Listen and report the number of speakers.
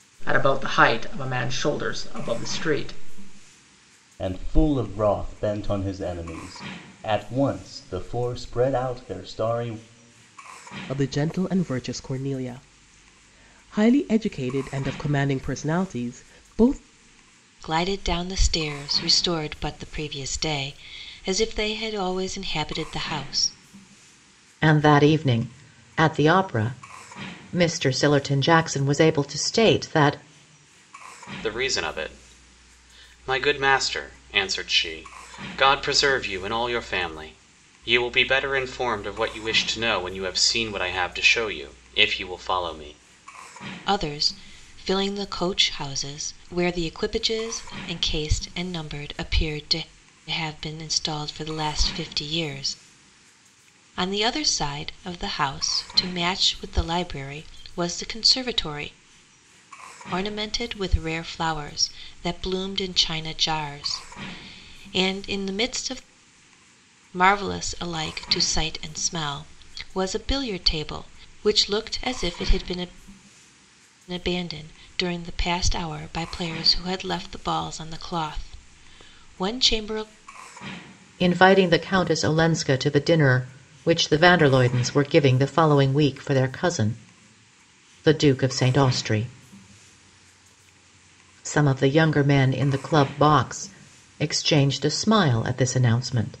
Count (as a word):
six